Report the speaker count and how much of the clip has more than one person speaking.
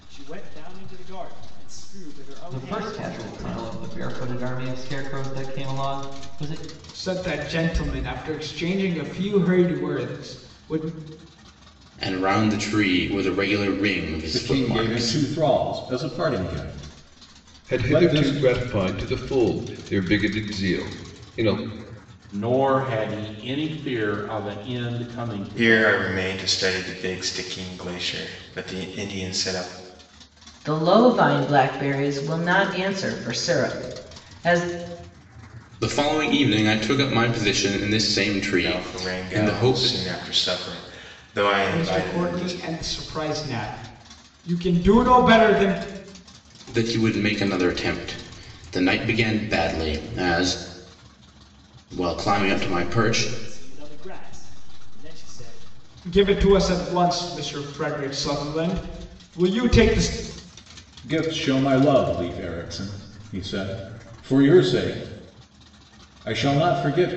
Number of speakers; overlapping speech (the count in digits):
9, about 10%